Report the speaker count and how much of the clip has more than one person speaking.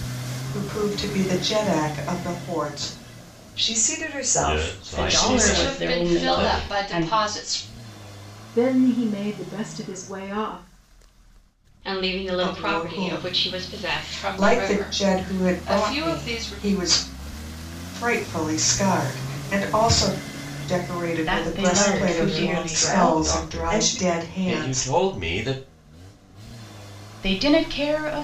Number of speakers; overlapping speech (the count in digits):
7, about 38%